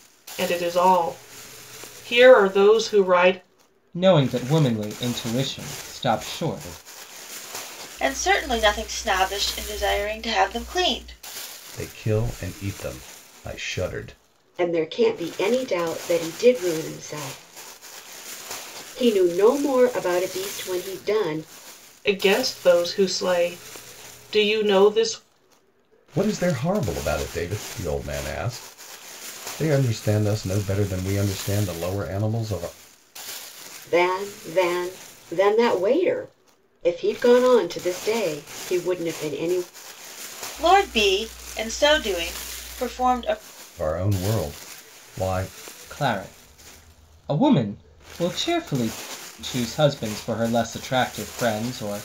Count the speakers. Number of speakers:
five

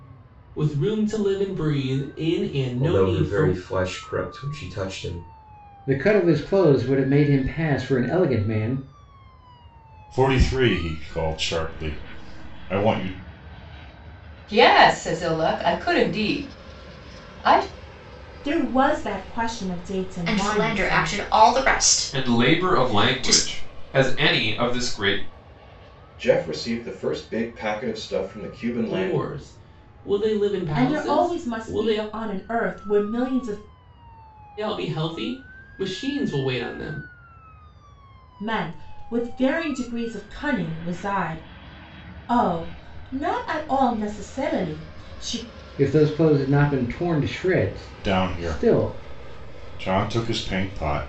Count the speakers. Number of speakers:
nine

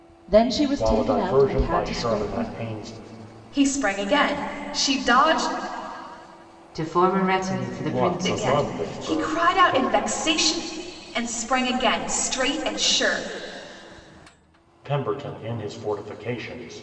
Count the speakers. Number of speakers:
four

